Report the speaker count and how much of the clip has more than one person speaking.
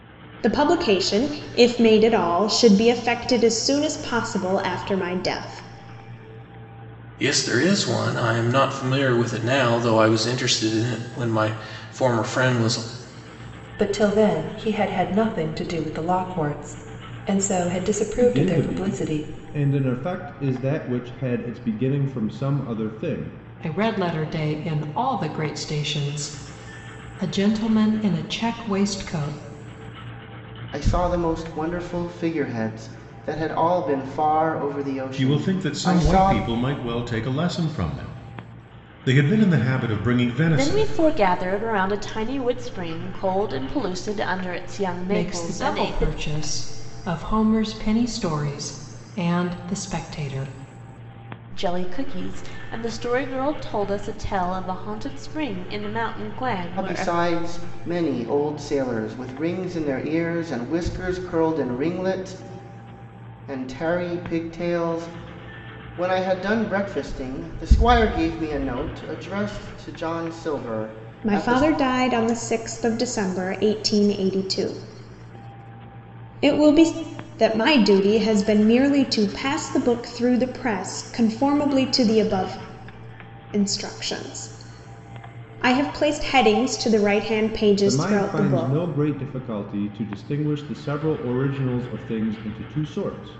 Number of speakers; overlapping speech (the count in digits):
8, about 6%